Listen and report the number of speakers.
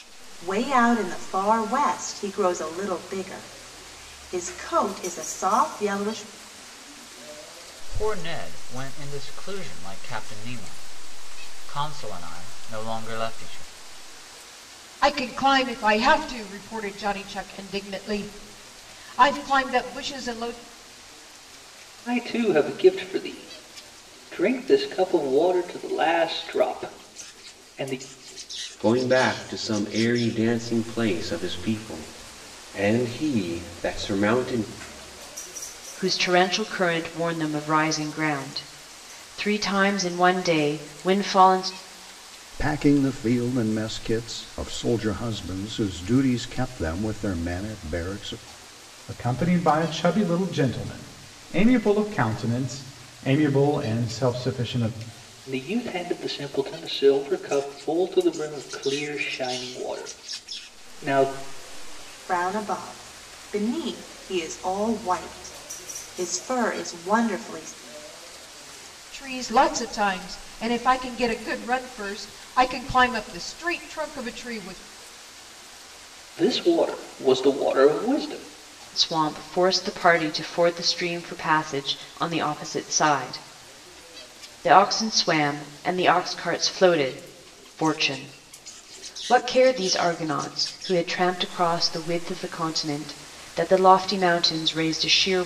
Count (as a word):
eight